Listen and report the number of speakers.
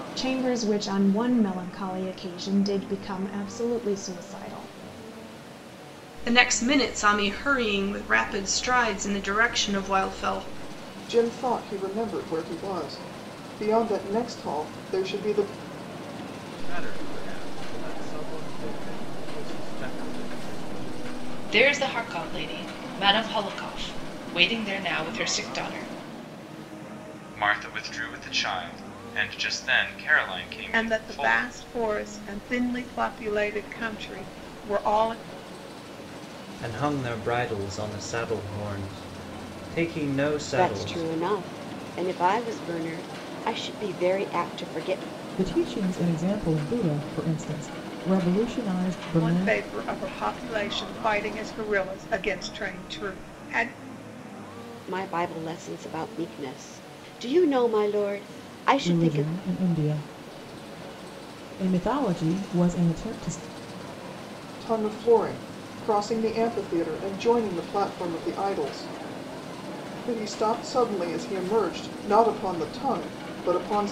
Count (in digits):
10